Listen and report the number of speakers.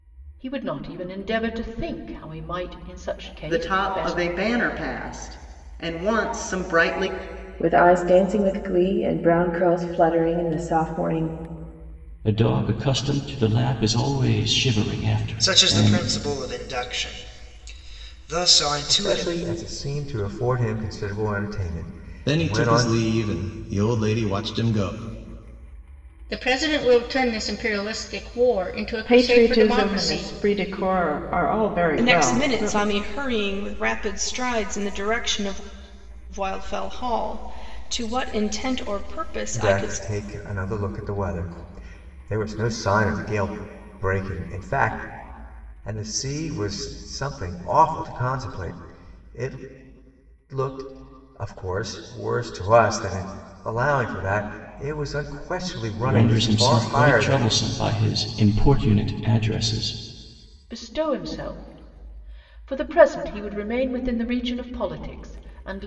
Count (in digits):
10